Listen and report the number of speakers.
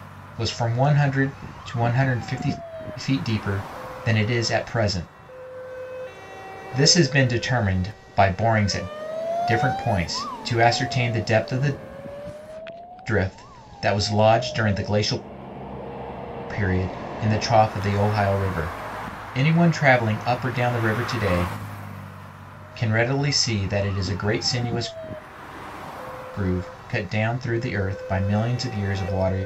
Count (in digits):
1